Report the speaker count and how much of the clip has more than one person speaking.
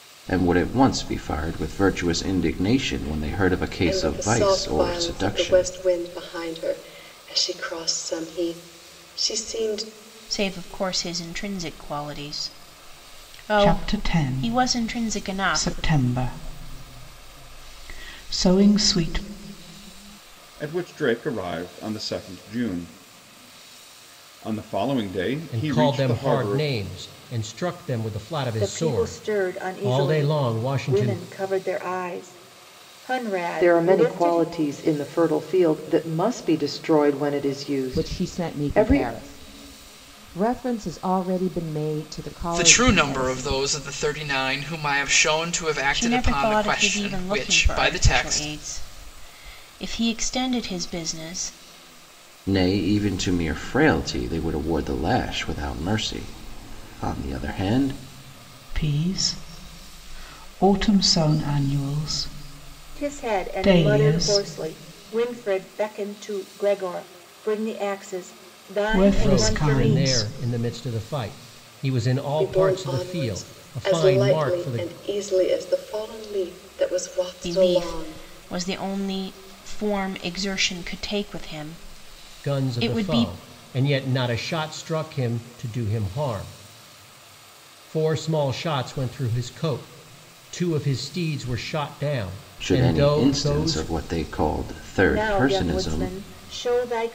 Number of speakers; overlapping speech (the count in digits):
10, about 24%